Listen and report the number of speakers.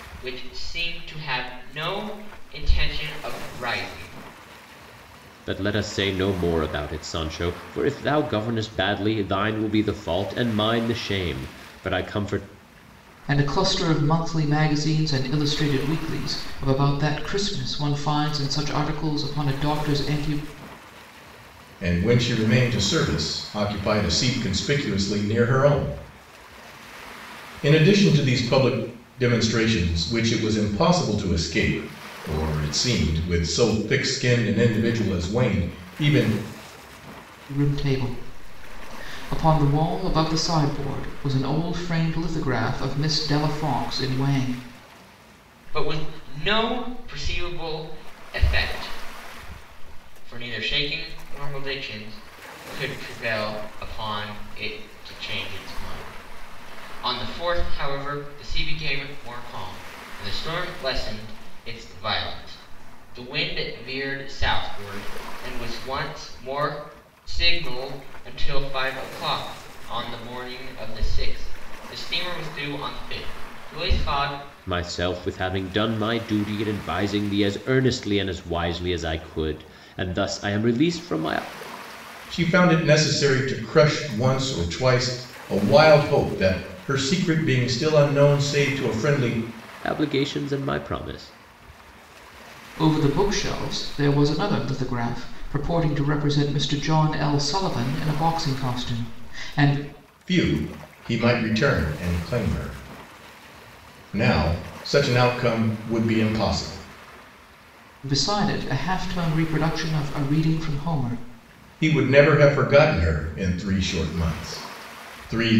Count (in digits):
4